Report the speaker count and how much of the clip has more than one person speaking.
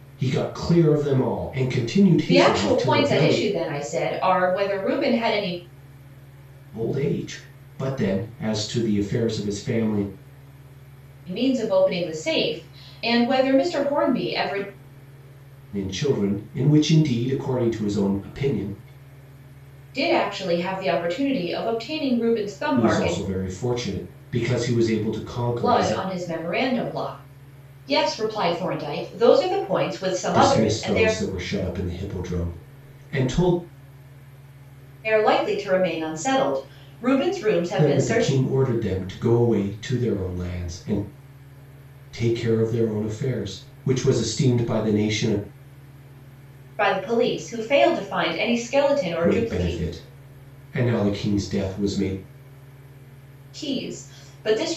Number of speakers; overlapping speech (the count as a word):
two, about 8%